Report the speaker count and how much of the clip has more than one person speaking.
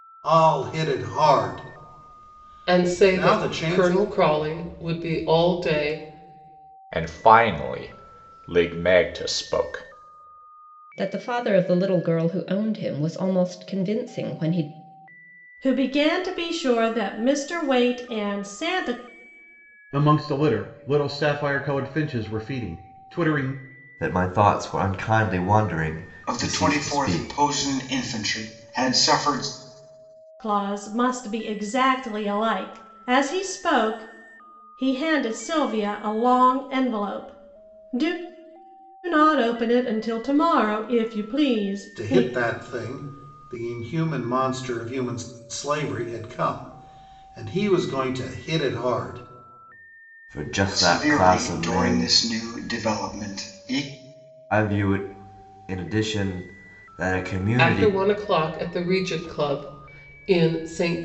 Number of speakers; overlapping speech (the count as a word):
eight, about 8%